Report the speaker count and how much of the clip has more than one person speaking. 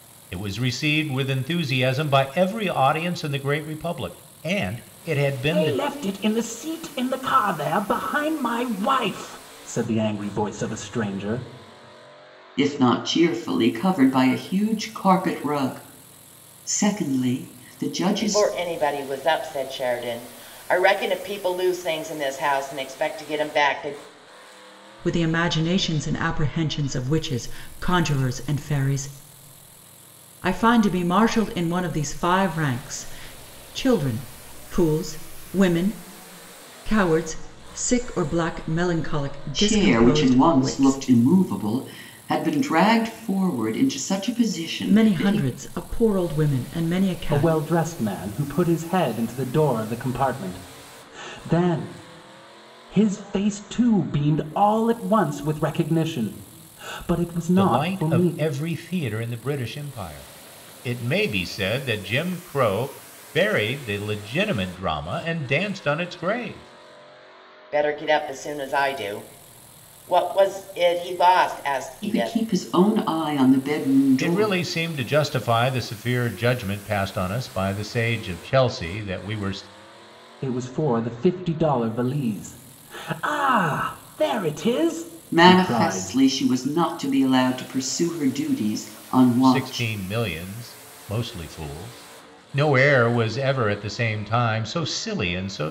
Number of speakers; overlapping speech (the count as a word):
five, about 6%